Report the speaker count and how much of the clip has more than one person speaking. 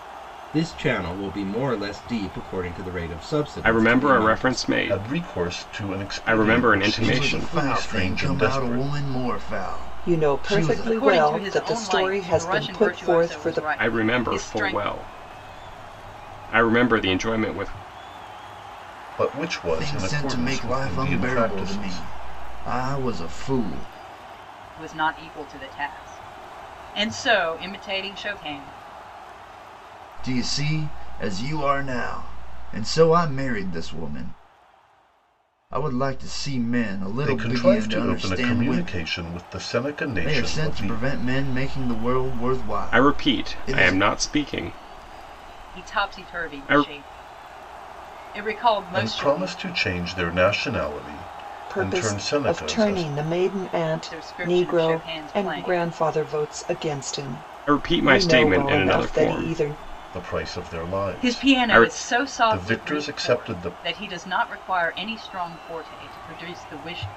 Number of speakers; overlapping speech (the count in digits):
6, about 41%